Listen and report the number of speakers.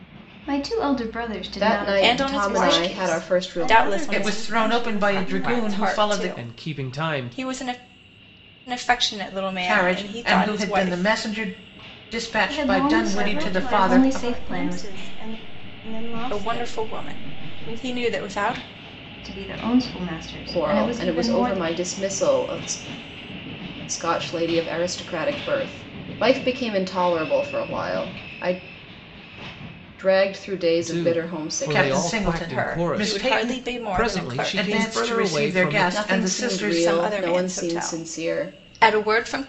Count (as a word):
six